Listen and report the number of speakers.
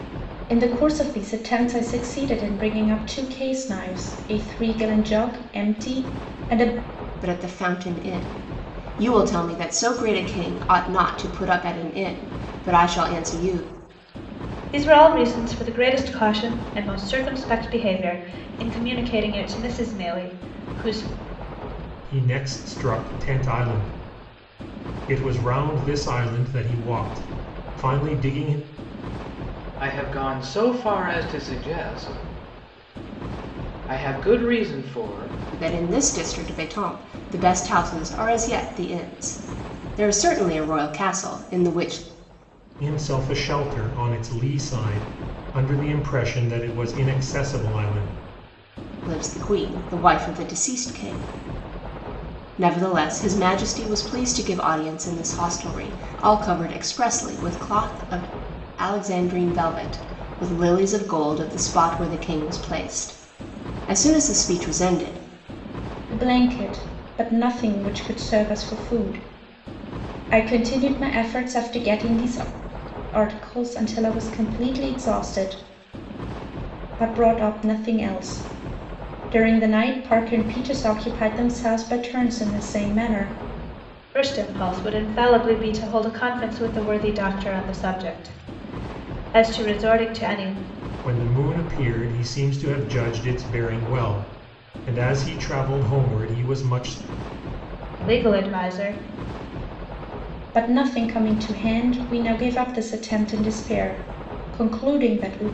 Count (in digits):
5